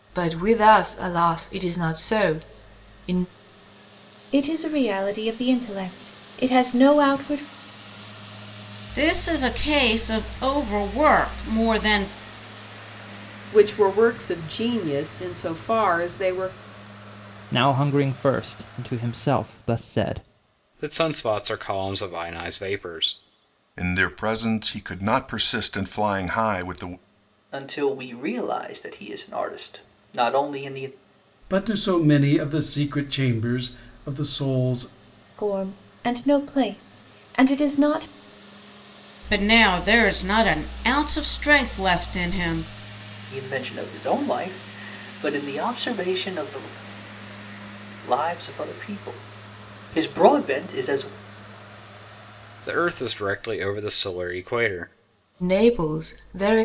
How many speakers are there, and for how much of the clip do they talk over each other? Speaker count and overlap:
9, no overlap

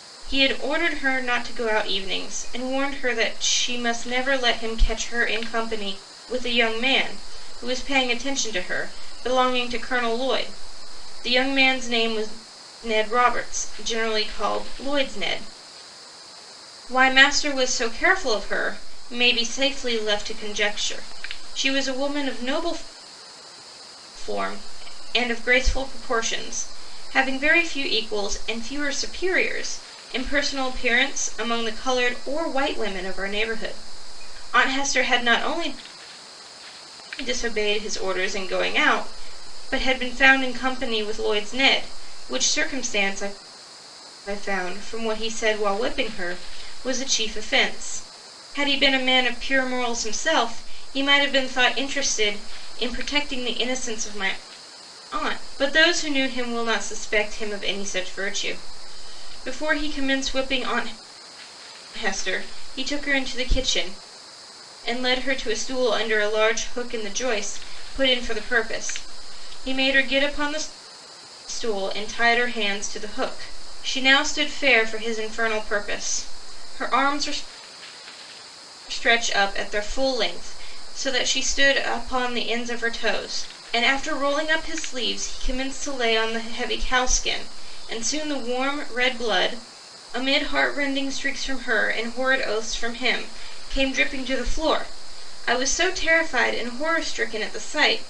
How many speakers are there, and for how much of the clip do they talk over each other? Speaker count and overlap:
1, no overlap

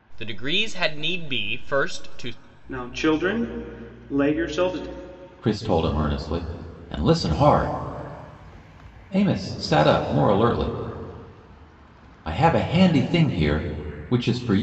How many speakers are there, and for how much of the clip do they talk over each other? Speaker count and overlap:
3, no overlap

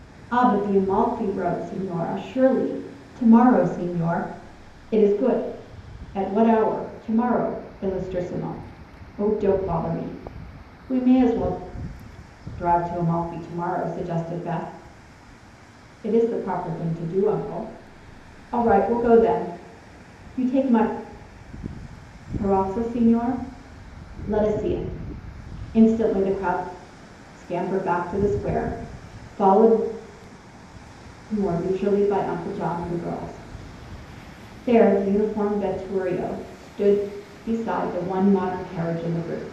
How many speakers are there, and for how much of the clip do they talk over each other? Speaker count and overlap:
1, no overlap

